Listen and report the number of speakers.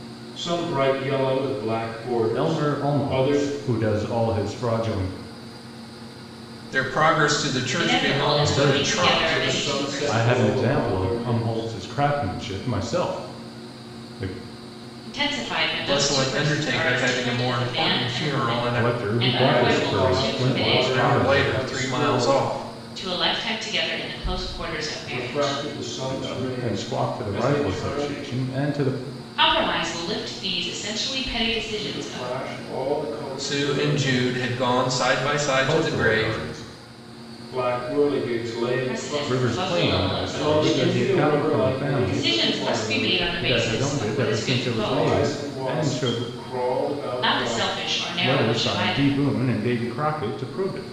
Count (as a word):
four